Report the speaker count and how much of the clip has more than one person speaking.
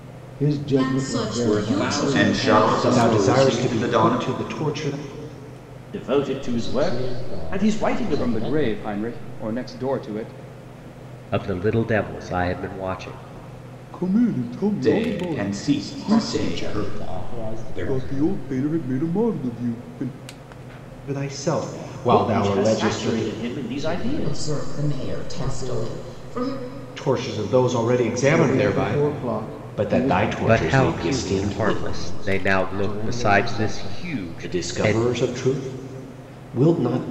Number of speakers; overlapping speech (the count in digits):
9, about 50%